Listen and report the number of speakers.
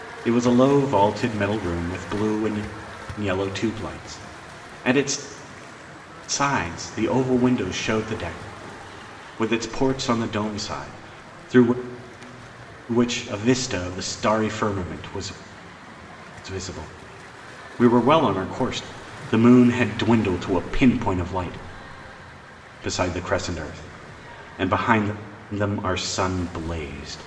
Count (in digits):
1